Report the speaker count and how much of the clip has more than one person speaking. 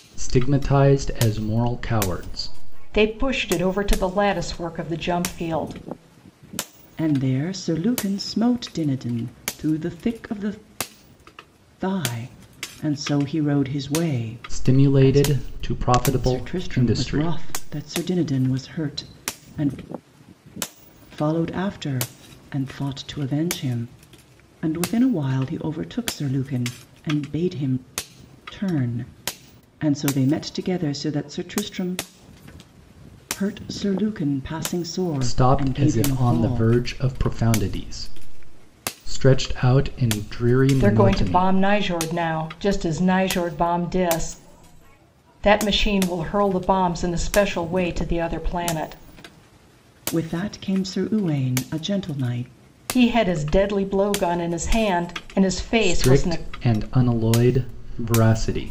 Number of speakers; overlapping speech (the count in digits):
3, about 8%